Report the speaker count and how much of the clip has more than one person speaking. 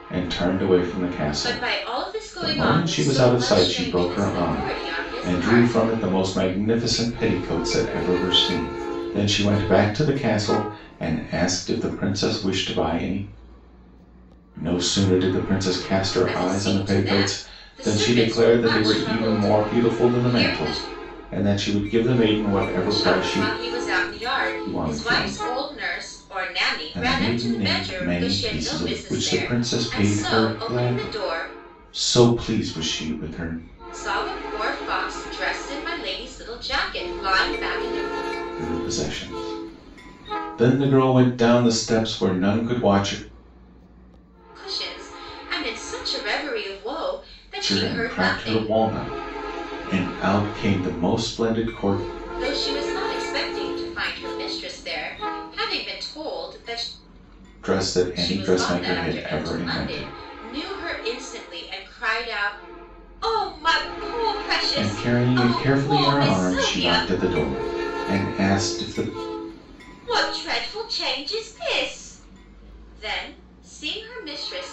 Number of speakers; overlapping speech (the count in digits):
2, about 29%